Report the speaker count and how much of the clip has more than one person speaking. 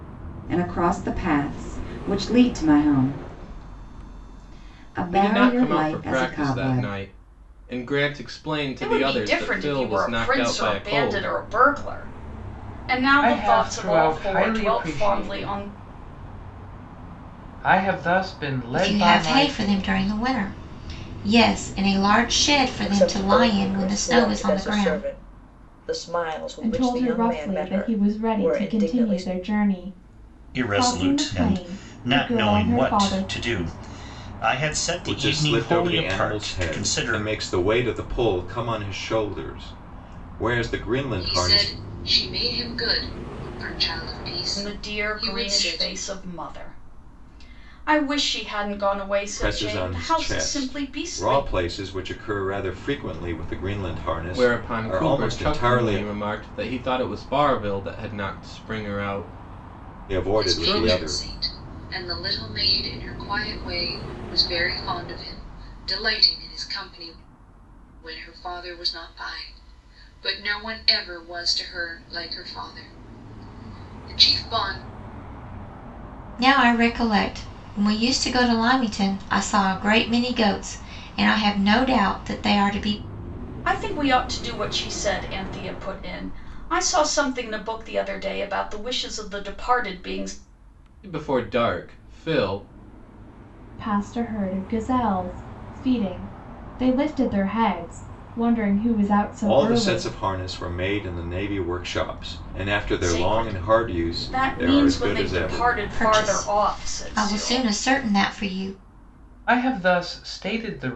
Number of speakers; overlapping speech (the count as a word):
ten, about 28%